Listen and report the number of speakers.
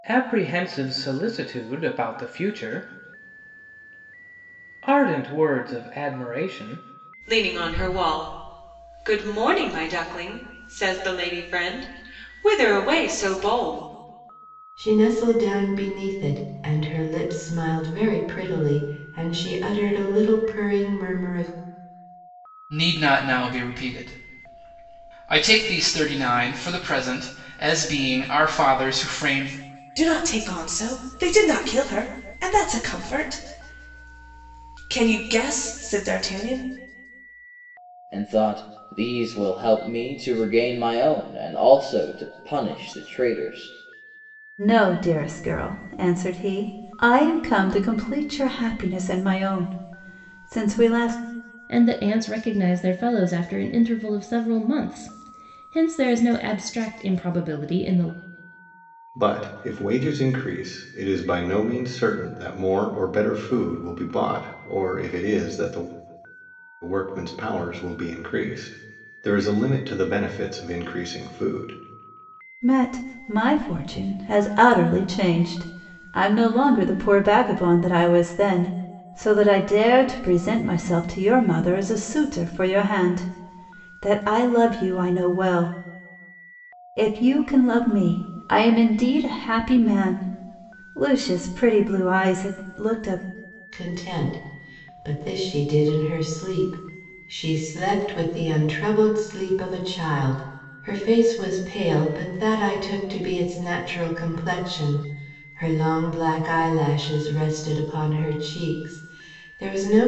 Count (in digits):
9